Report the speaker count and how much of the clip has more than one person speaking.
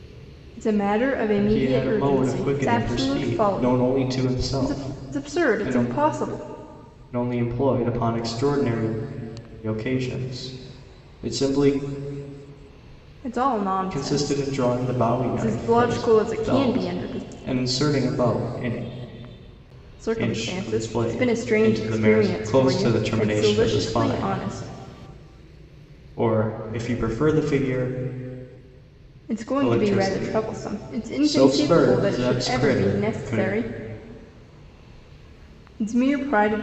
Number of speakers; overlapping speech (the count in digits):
2, about 42%